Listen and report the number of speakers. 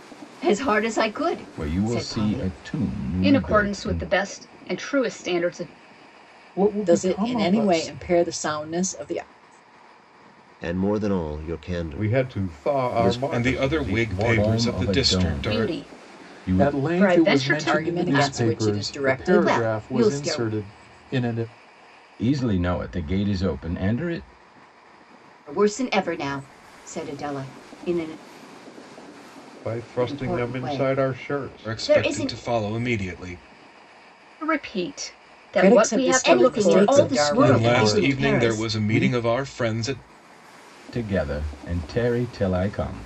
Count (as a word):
eight